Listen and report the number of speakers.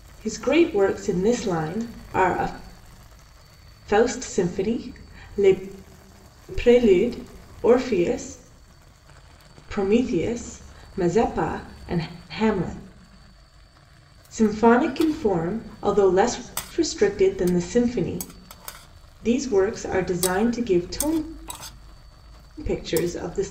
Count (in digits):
1